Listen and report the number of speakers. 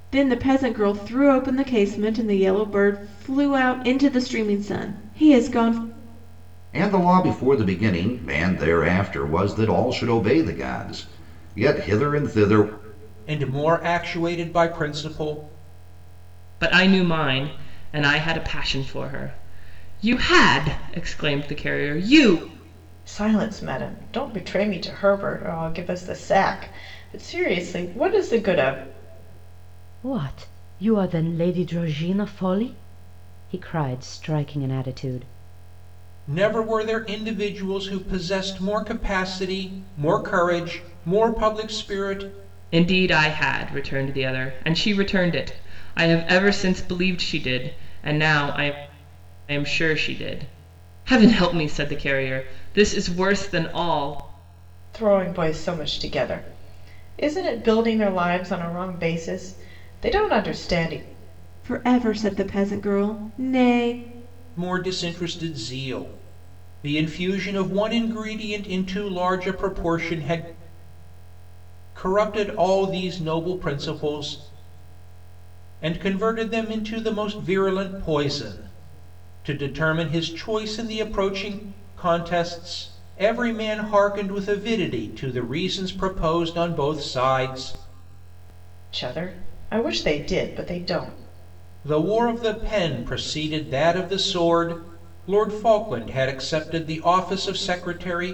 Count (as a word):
six